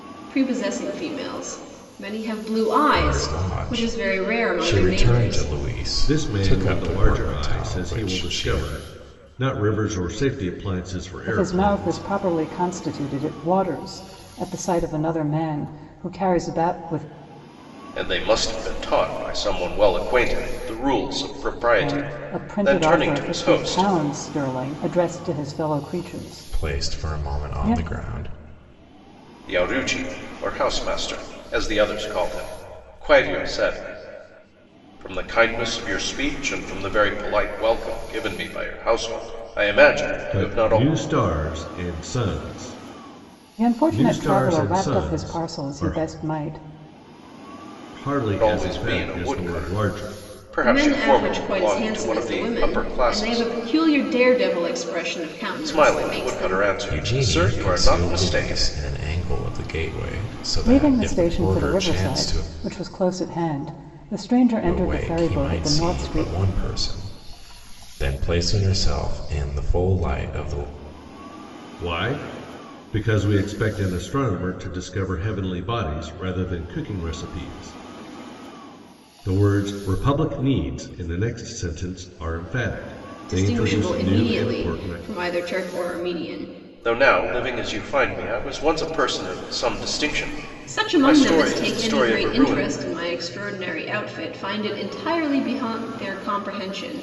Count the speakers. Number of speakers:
five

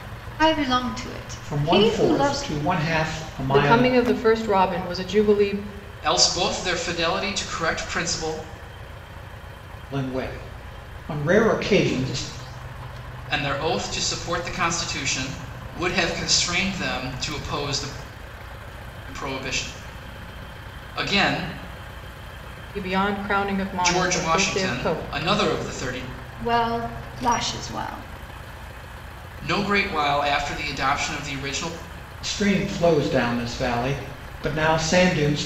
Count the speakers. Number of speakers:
four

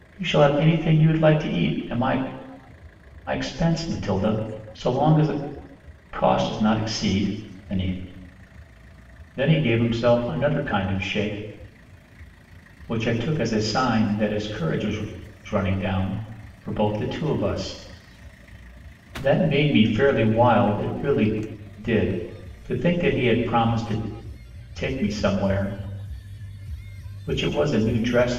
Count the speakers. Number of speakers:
one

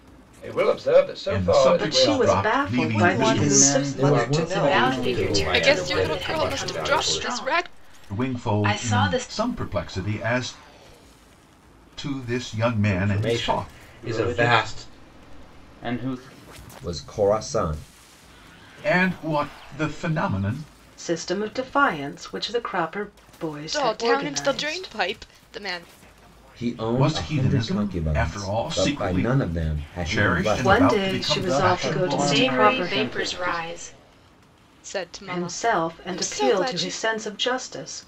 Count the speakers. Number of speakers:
nine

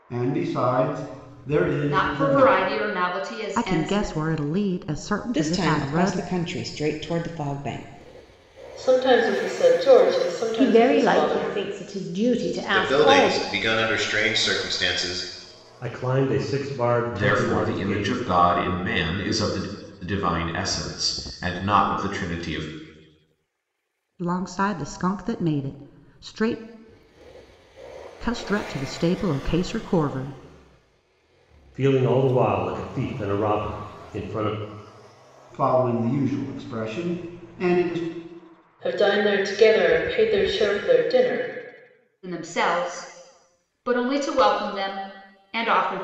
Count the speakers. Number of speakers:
nine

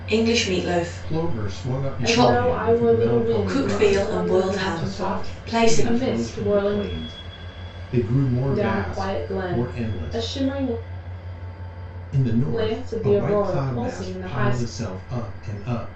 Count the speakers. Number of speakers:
three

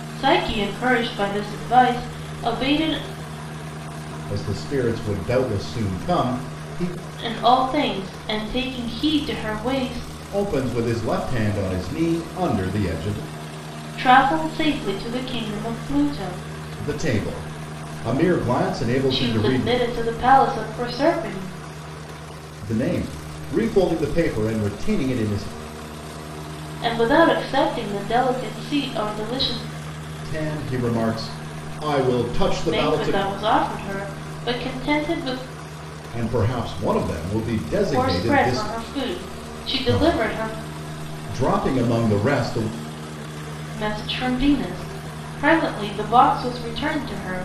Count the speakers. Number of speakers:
two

